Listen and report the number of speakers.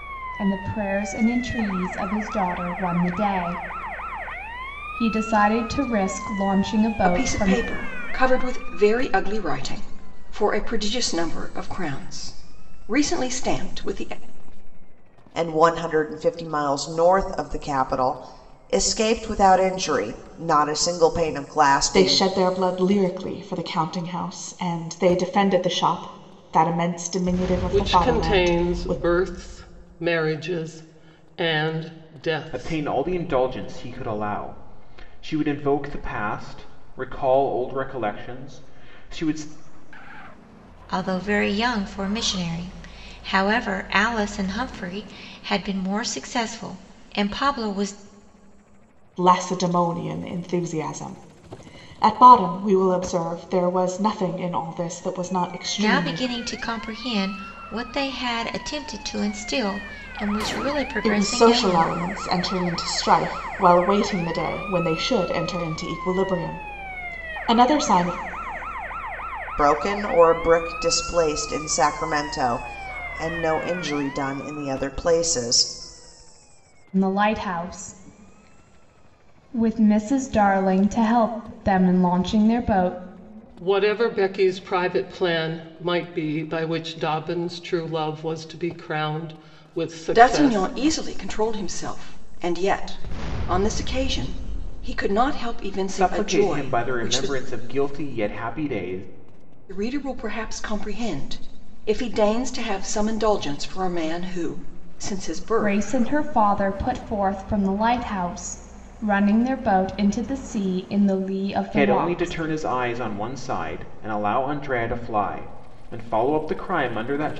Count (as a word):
seven